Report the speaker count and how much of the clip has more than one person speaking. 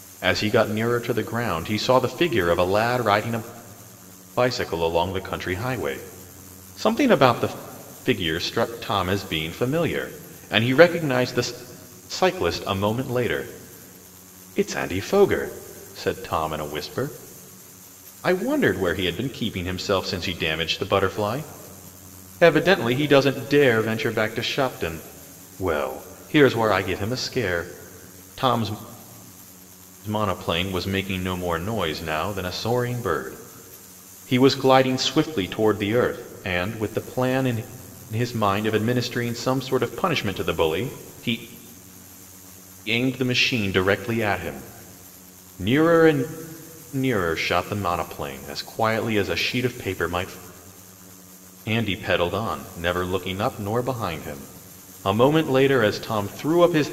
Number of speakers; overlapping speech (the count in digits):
1, no overlap